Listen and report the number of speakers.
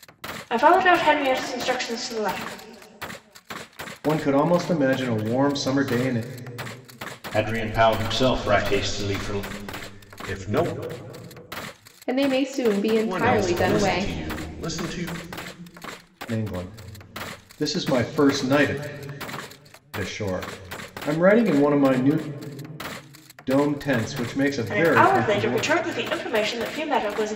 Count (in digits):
5